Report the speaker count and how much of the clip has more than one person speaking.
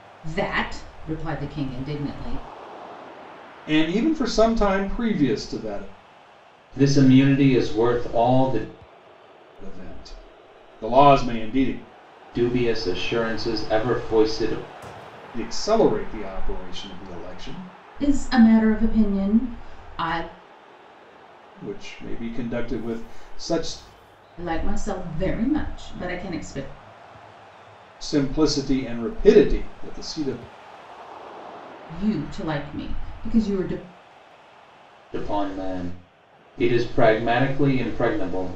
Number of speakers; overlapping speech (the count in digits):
3, no overlap